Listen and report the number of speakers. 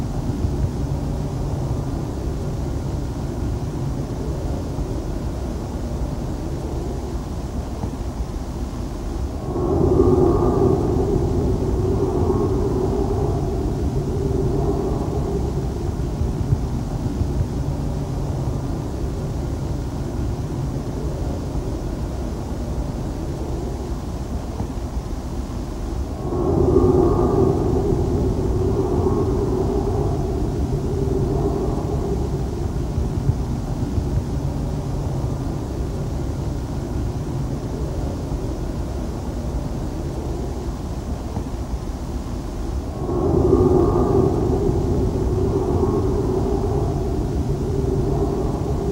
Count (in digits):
0